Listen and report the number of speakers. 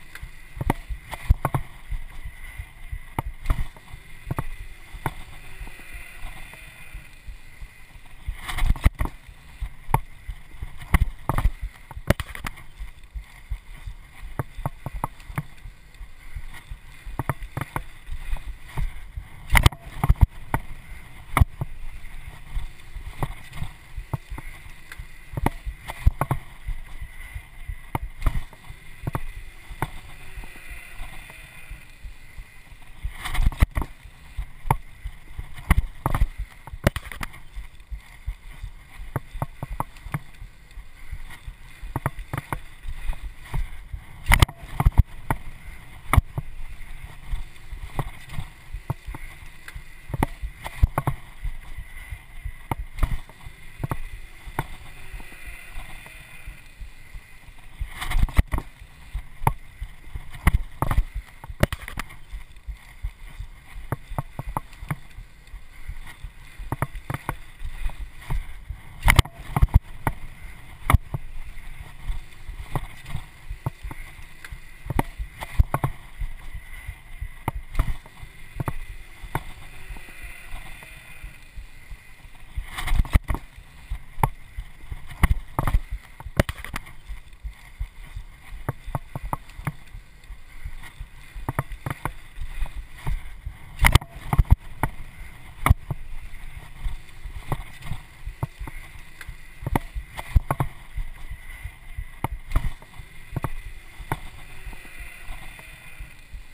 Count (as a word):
zero